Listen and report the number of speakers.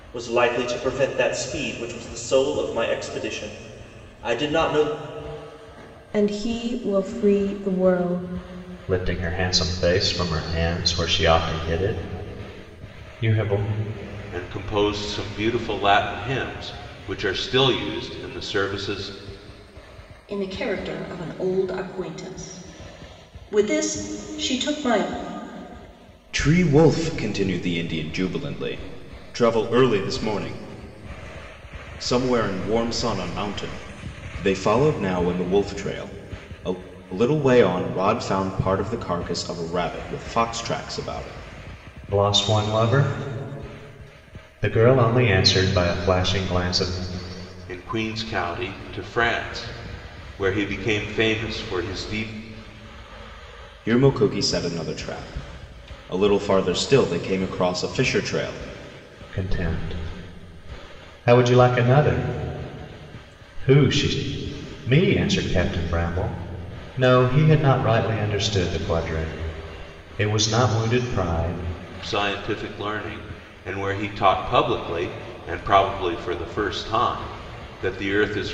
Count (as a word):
six